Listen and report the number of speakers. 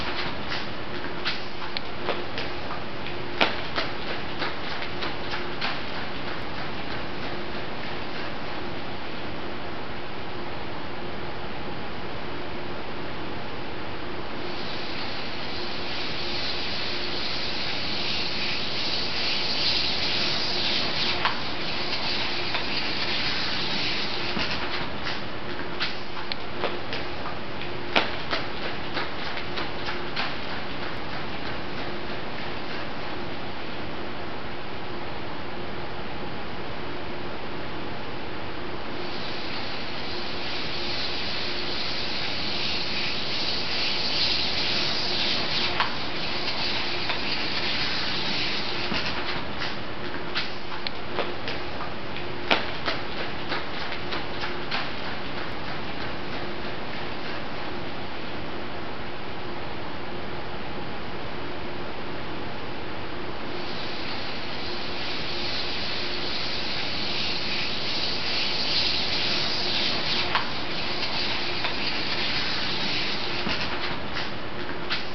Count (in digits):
0